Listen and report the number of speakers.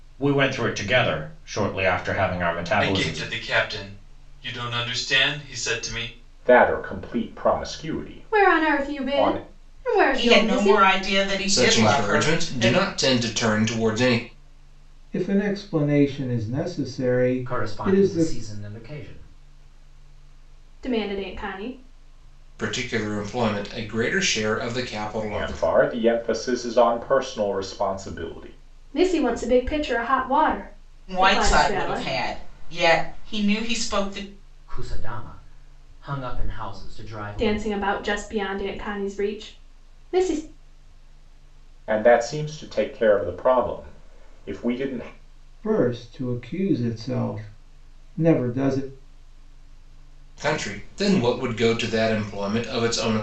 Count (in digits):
8